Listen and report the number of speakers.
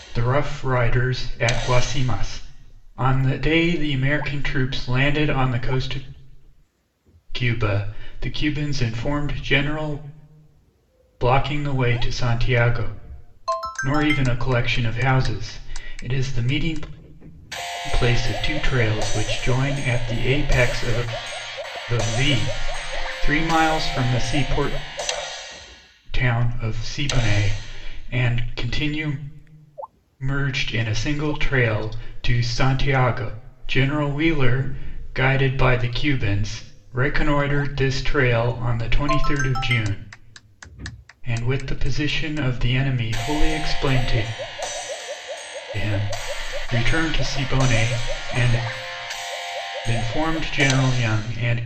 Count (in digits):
1